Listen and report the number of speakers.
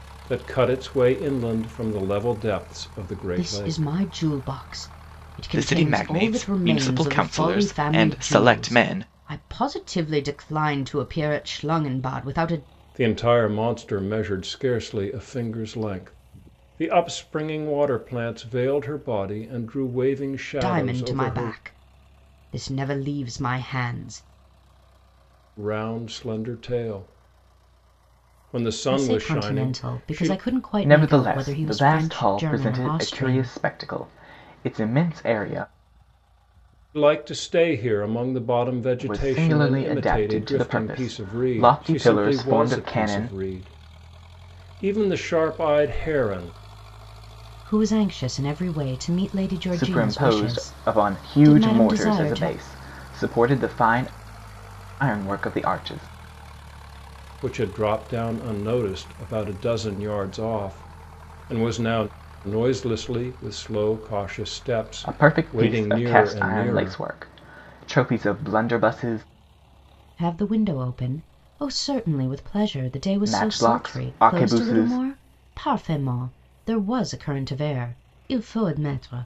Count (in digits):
3